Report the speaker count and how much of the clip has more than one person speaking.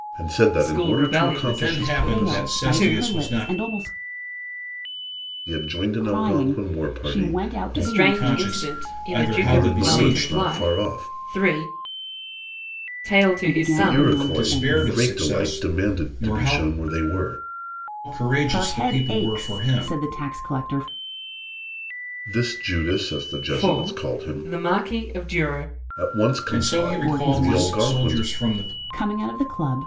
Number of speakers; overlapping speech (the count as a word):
four, about 54%